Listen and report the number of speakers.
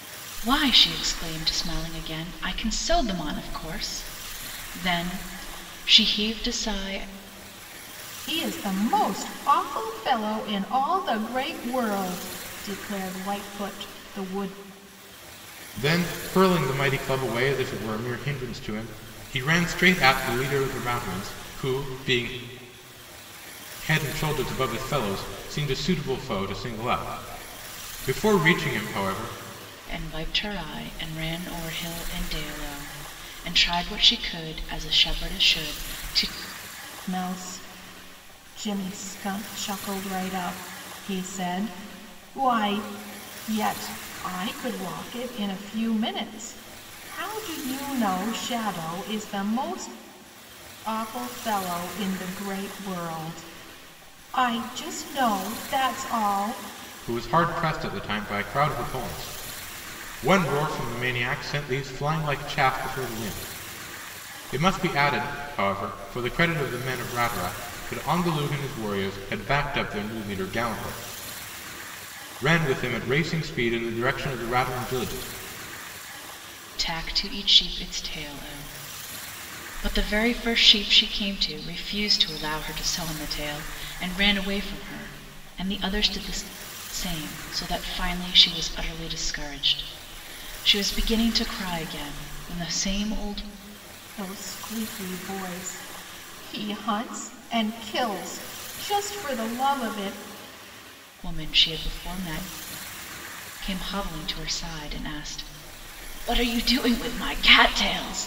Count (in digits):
3